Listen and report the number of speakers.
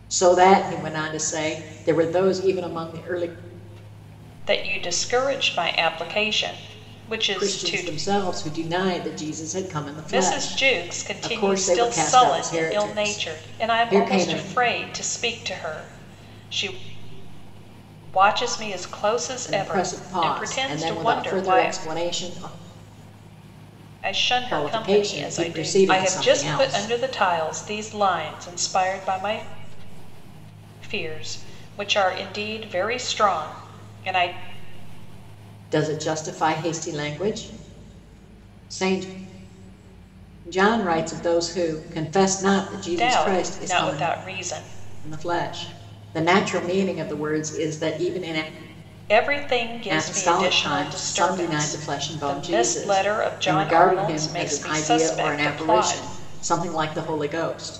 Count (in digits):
2